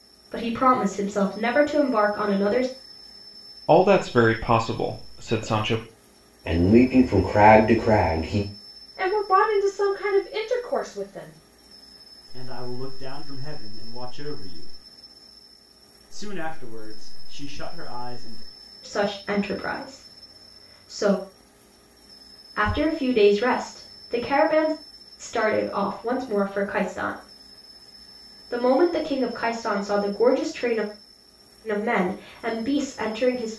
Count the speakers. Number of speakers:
5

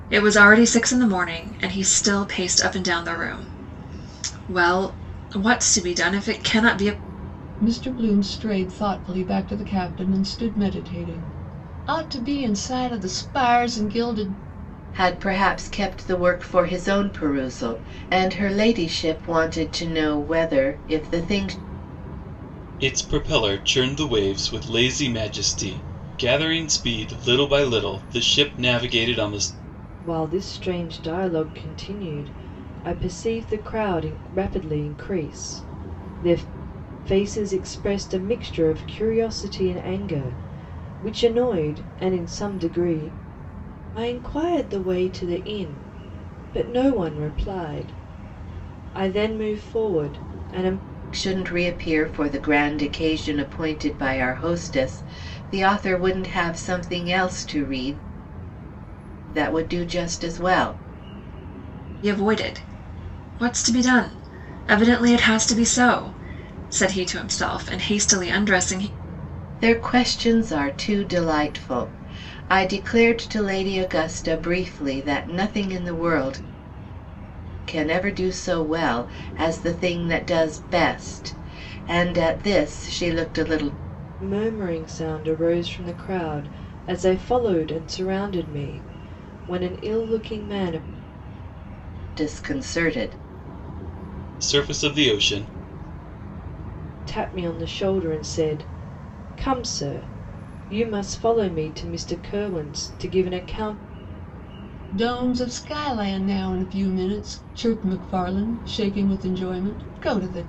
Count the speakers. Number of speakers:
5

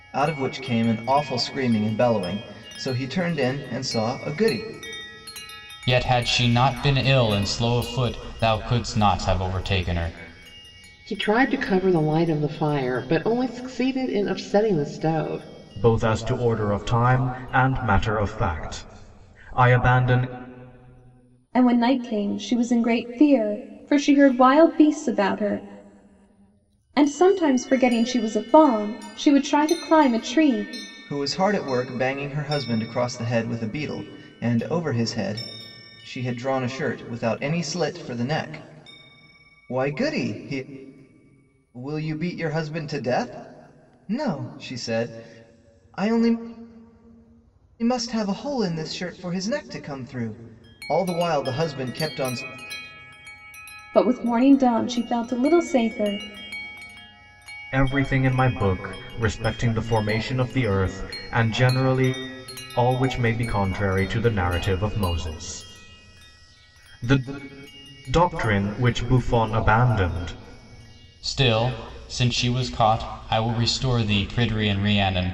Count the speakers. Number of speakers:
5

